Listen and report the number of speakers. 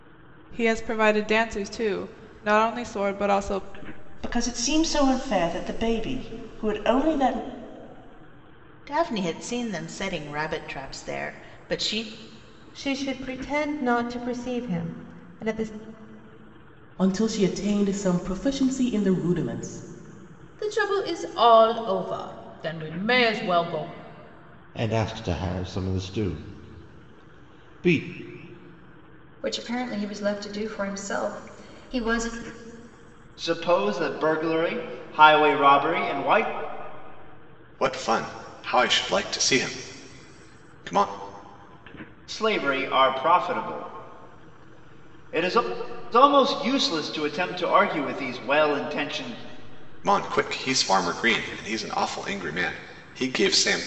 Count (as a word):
ten